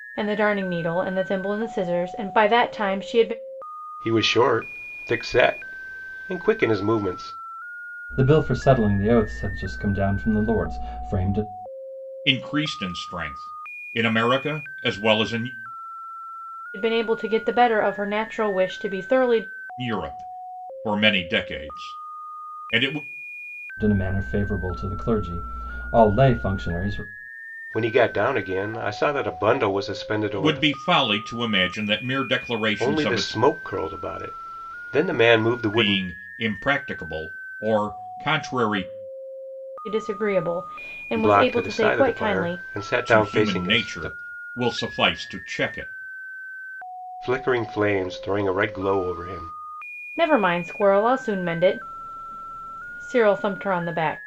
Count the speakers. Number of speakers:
four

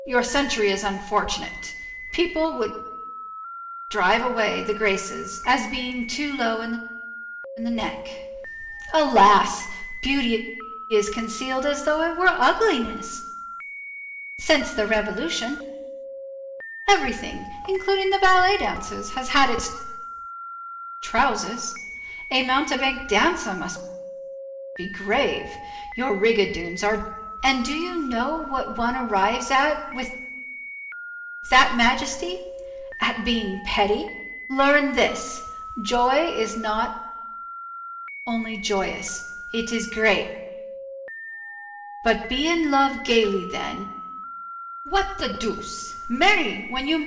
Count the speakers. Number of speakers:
one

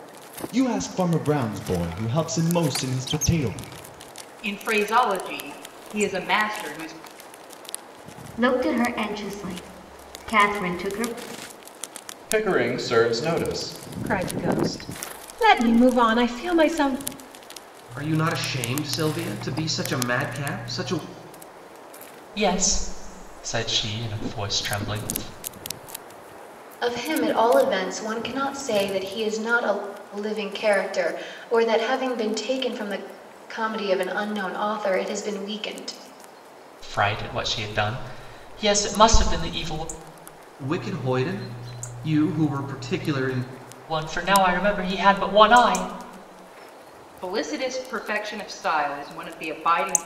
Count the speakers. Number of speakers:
eight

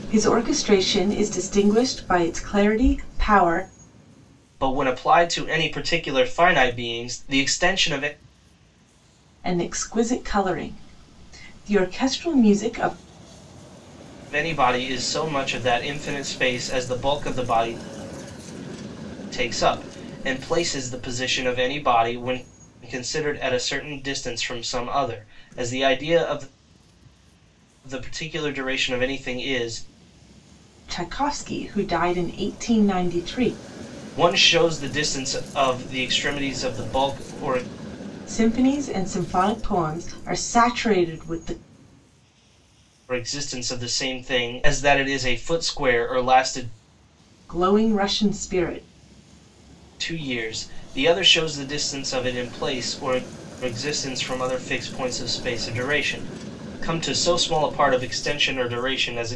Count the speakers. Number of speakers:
two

